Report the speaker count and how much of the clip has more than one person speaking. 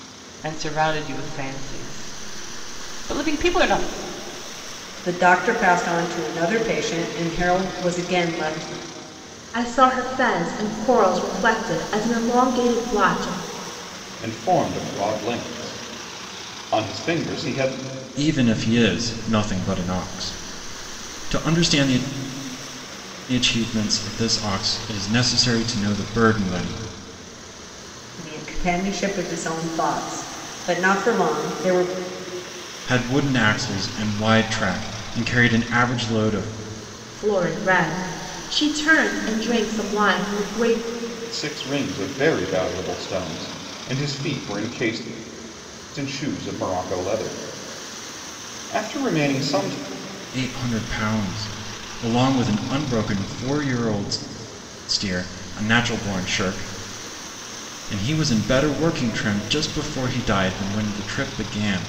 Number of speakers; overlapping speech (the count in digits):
5, no overlap